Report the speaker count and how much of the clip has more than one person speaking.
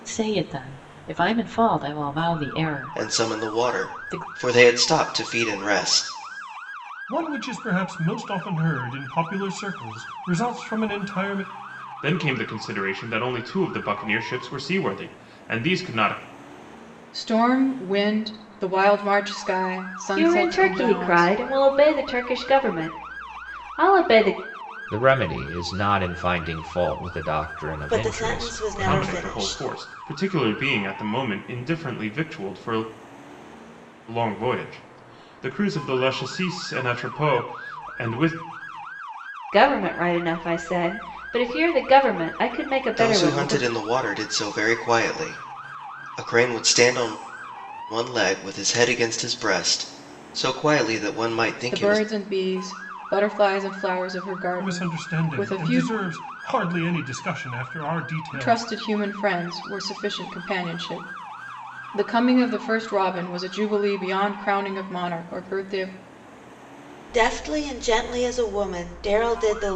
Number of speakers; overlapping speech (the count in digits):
8, about 10%